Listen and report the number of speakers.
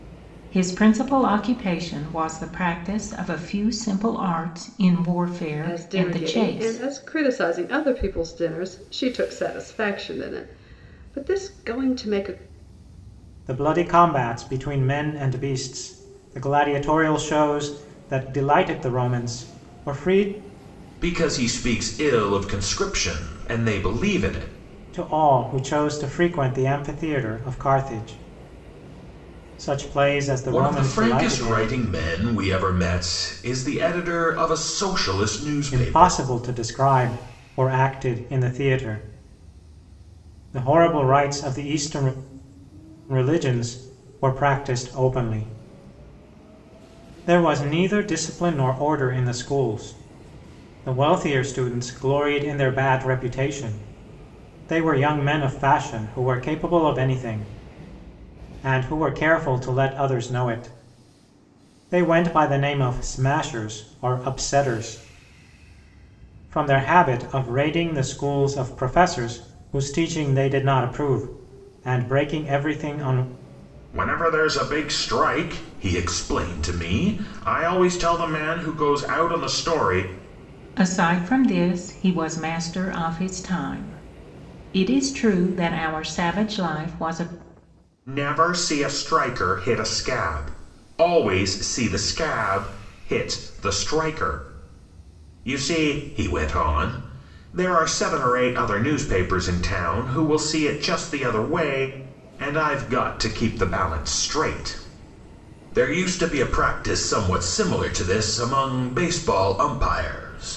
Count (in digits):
4